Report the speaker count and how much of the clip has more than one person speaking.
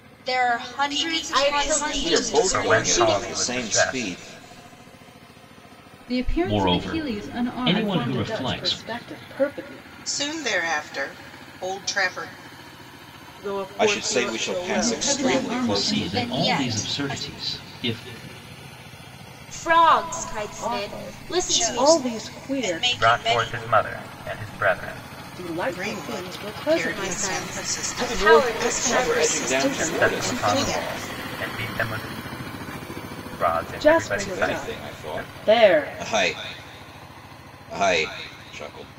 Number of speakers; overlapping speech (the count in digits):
10, about 51%